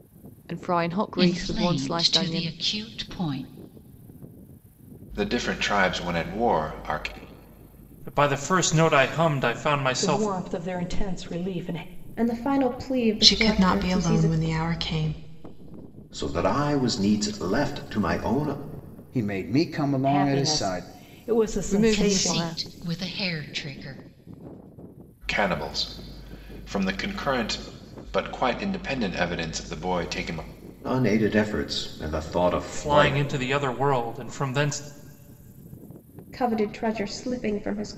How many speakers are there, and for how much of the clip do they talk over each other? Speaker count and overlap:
nine, about 14%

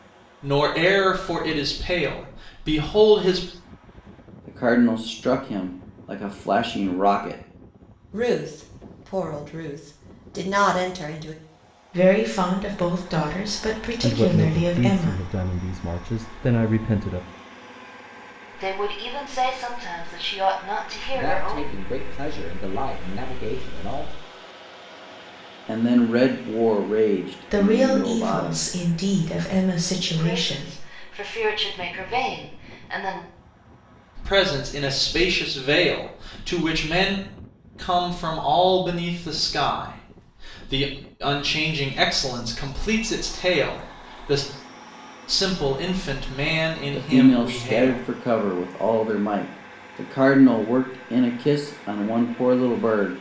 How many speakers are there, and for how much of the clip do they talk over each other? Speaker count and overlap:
seven, about 9%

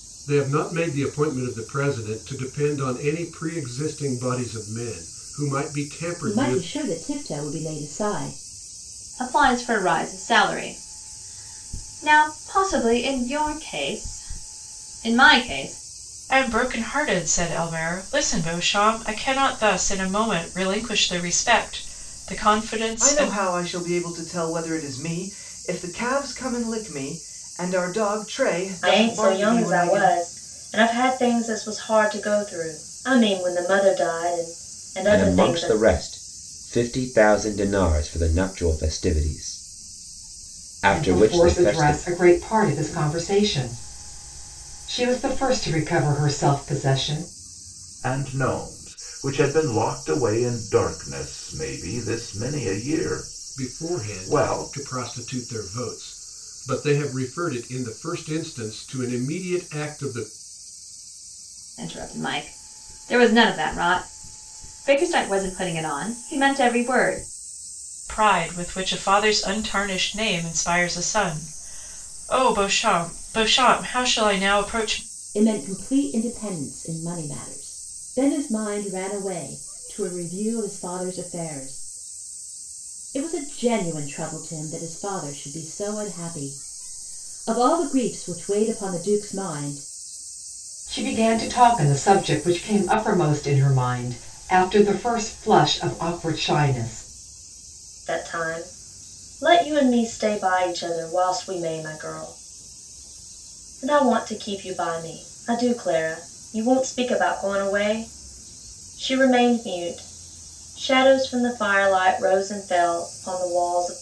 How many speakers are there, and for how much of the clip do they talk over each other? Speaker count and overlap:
nine, about 5%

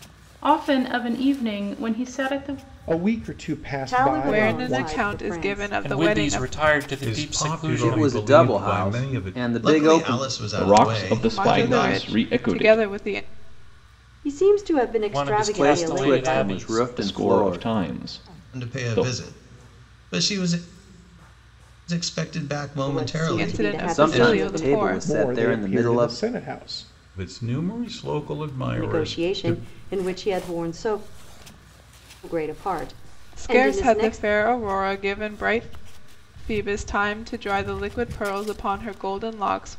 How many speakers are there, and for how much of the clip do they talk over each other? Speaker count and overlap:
nine, about 41%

